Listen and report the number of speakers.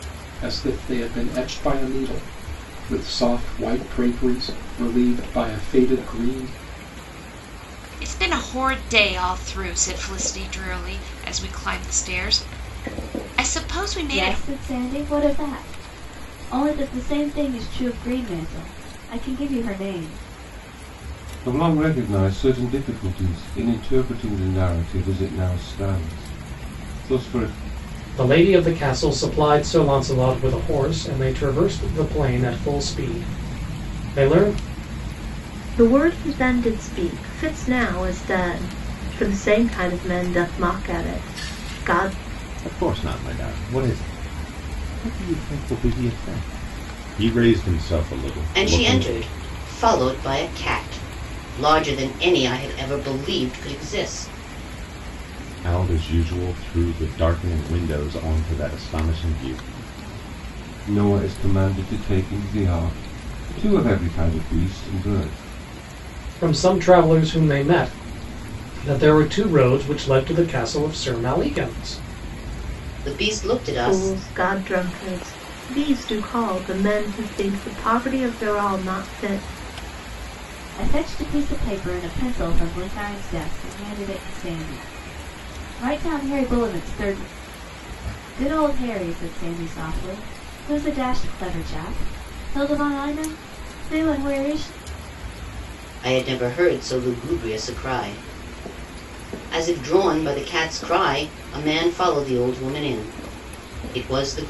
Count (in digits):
8